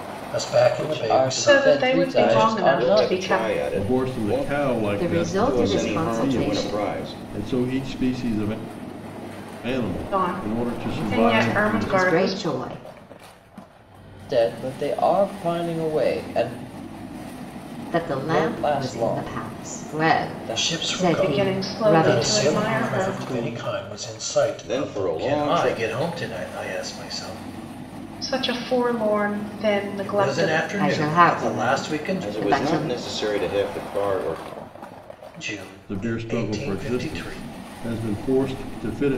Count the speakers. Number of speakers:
6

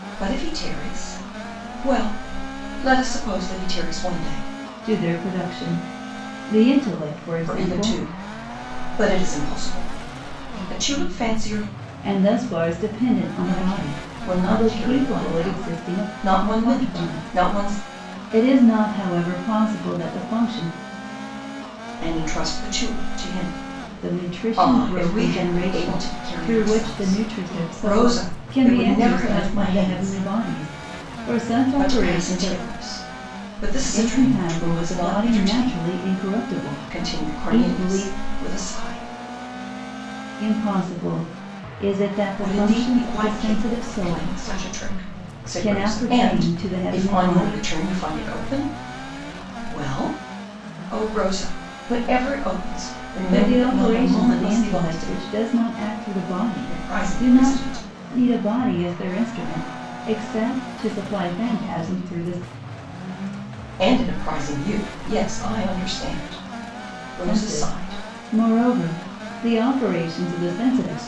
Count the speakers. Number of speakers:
2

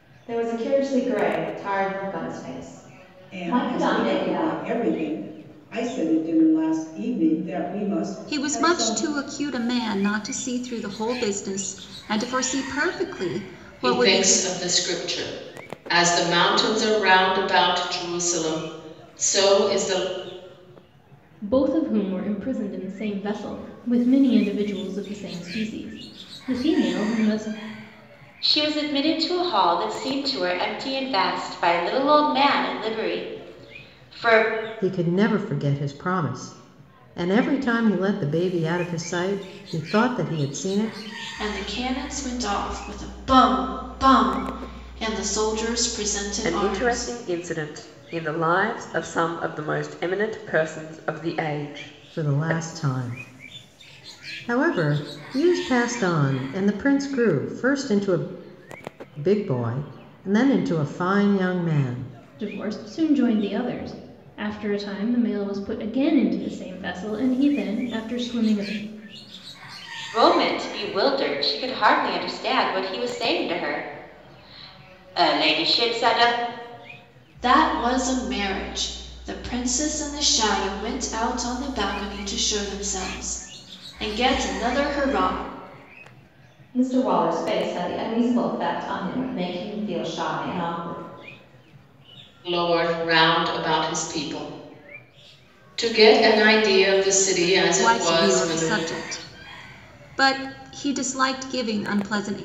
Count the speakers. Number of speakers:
9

